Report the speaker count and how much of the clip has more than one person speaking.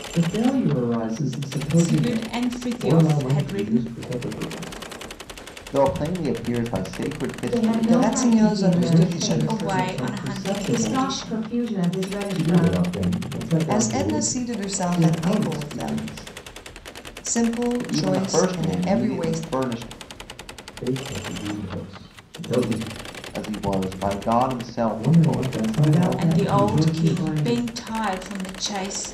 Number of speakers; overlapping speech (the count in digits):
6, about 43%